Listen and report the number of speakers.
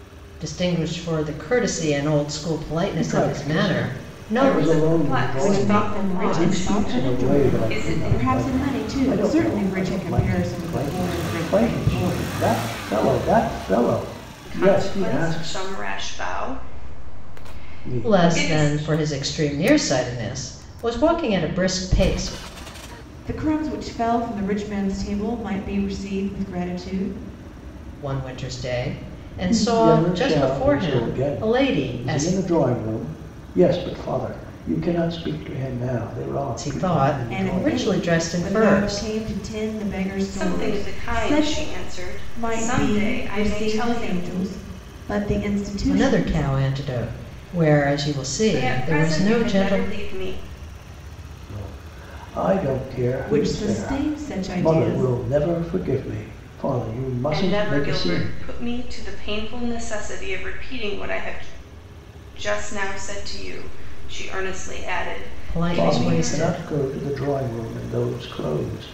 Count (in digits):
4